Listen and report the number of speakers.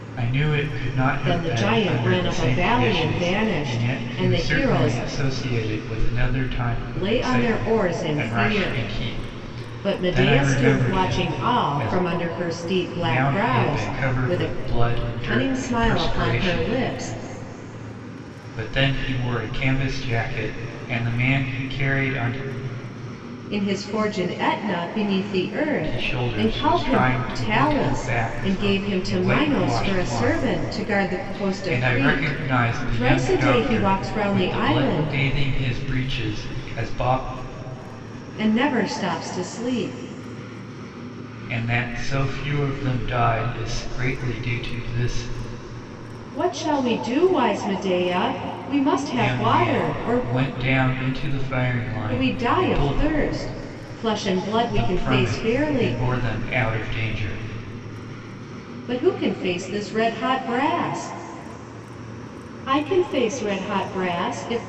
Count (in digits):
2